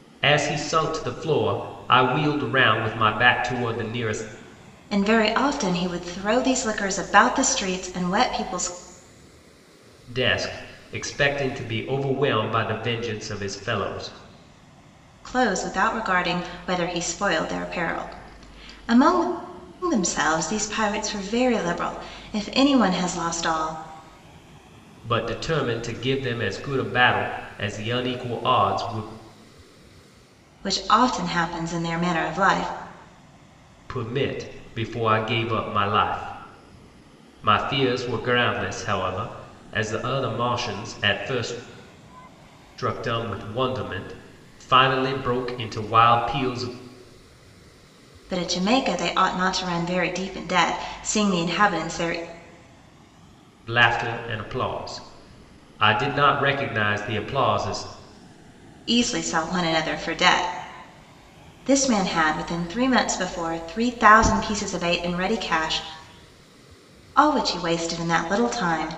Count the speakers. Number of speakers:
two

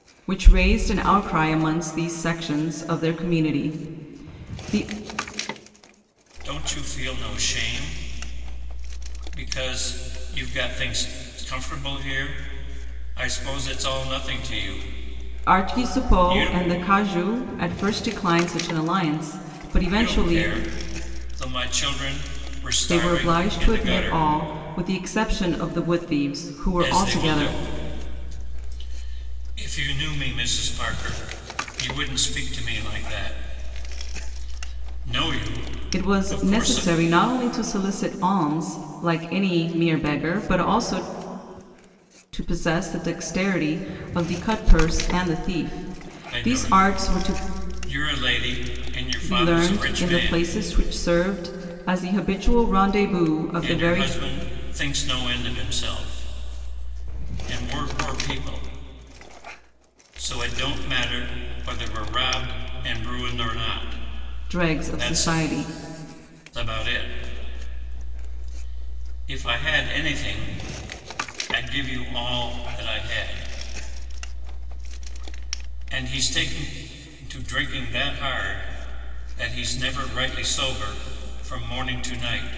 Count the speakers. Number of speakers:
two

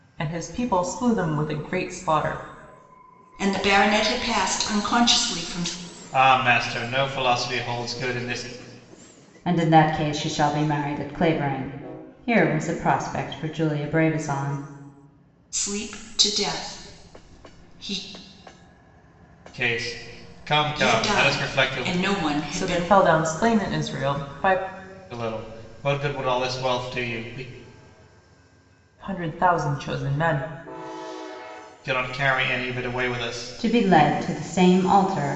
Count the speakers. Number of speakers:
four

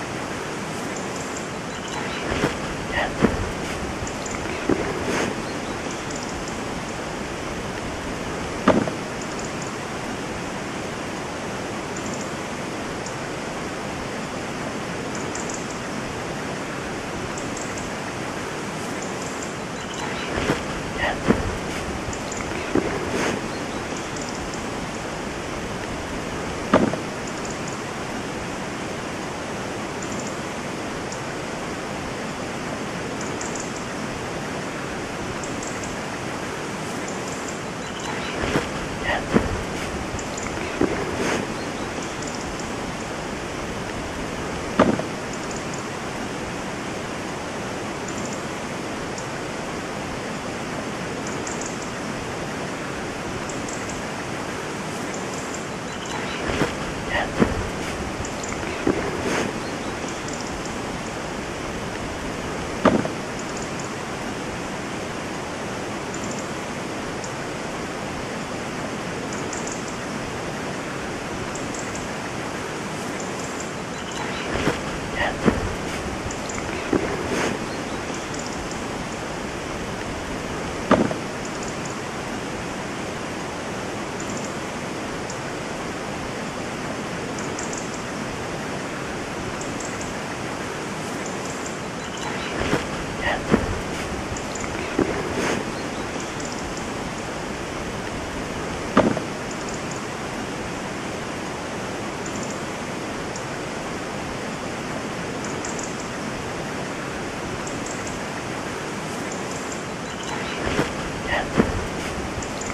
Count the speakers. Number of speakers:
zero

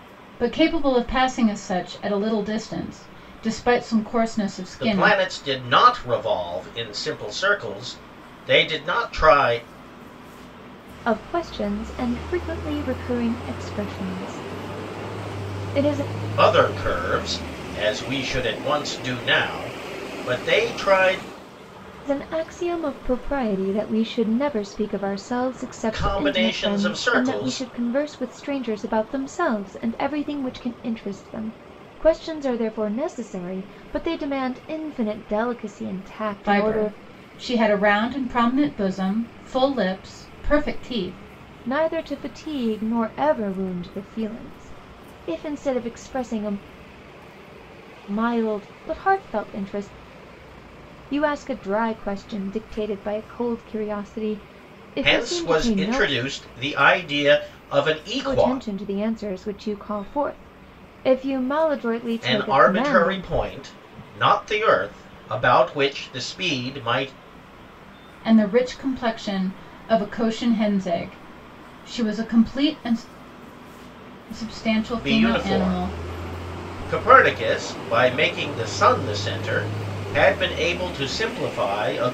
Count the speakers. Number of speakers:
three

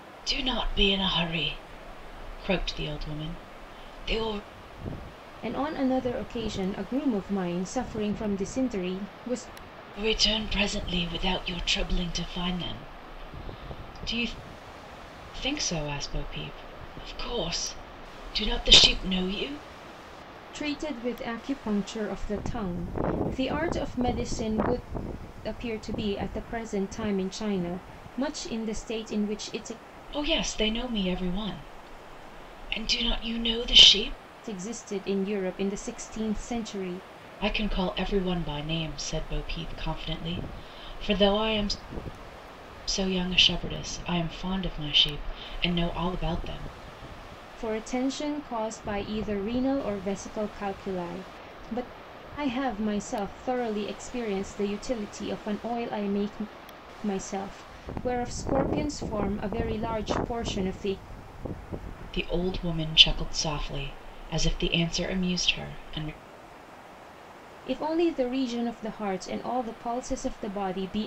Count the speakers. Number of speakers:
two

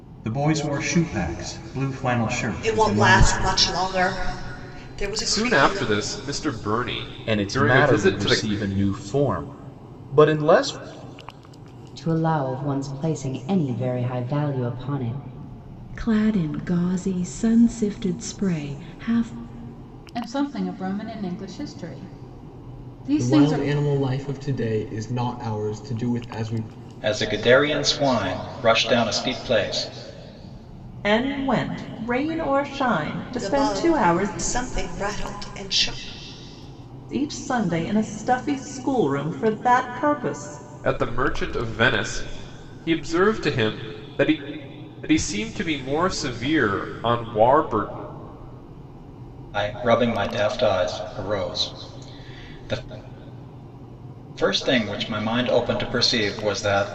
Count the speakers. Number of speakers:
ten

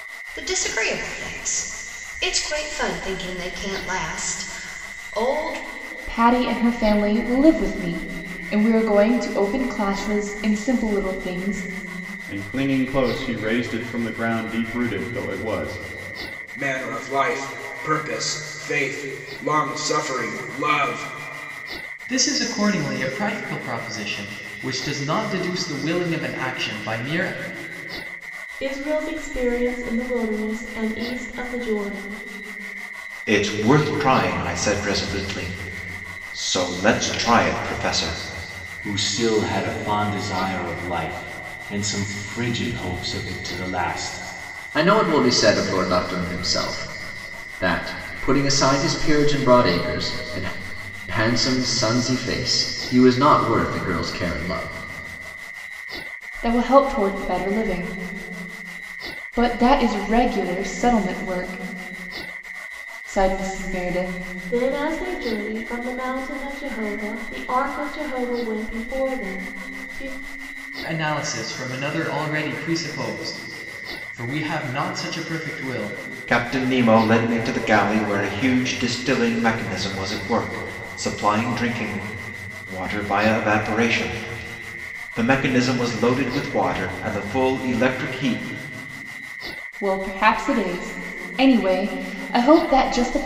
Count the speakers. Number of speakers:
nine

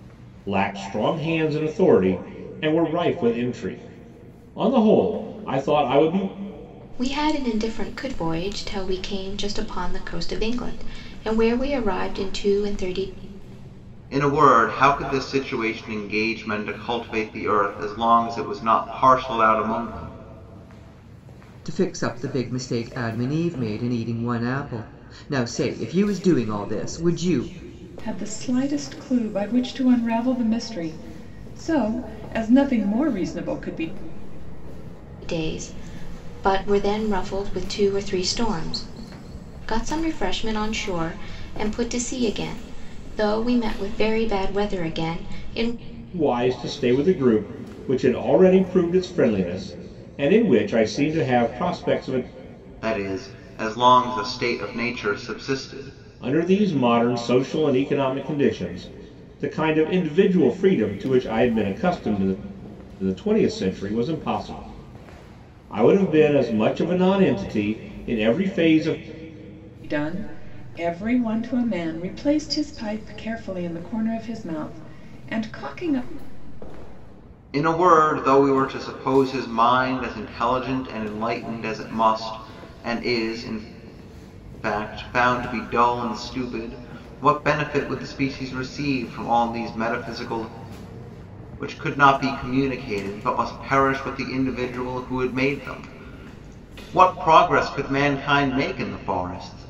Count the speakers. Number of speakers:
five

